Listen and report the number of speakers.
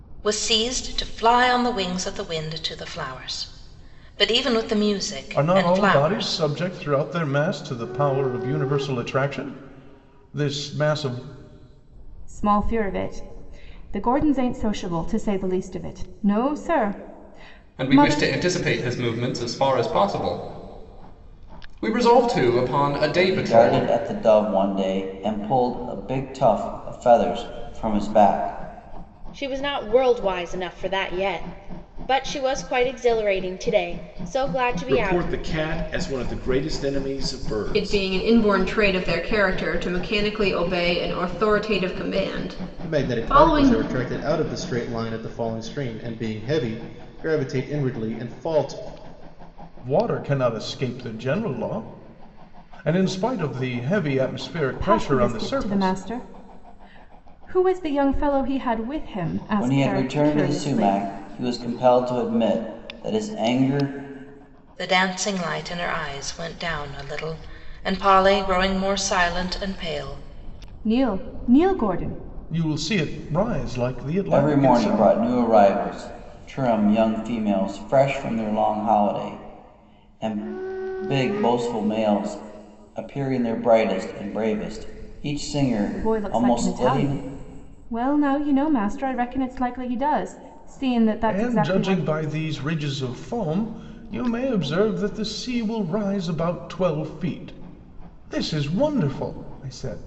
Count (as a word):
nine